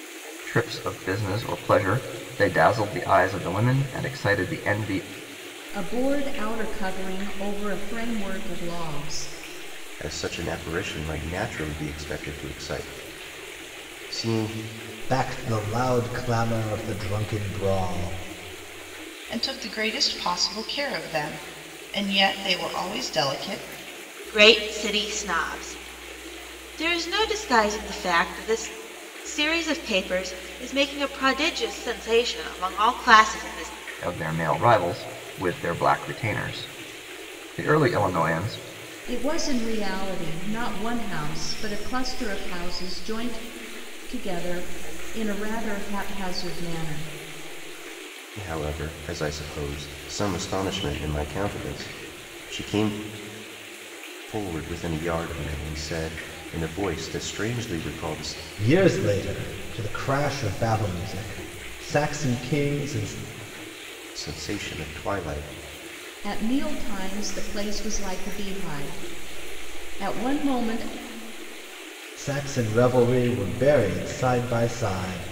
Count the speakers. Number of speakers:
6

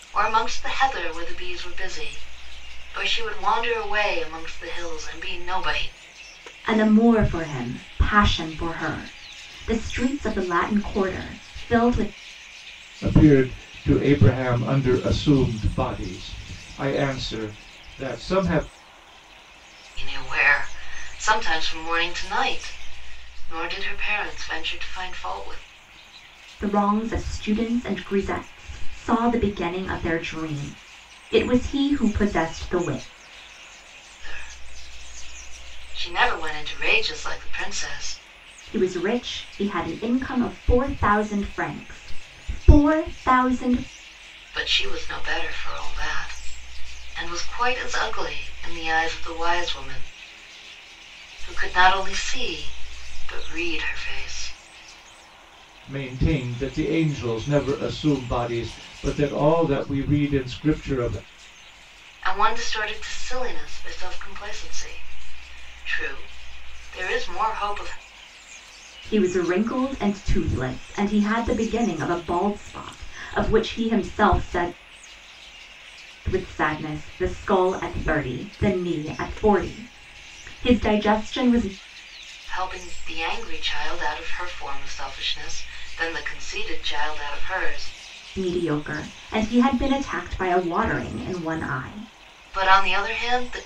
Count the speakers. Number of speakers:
3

